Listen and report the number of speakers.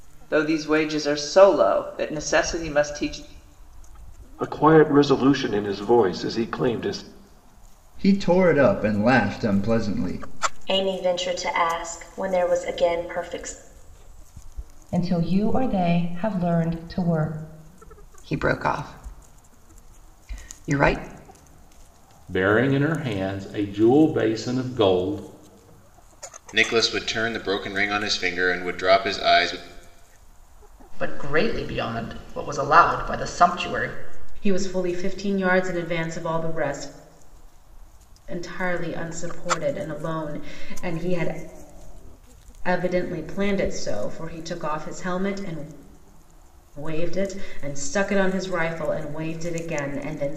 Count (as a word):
ten